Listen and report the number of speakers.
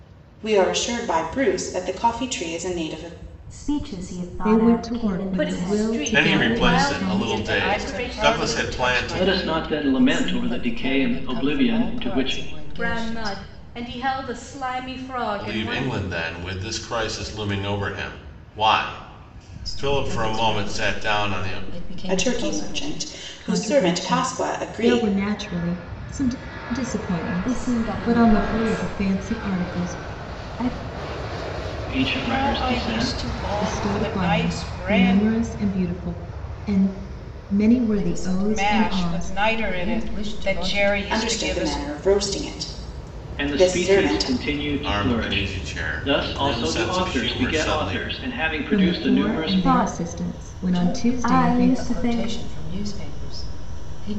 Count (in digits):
8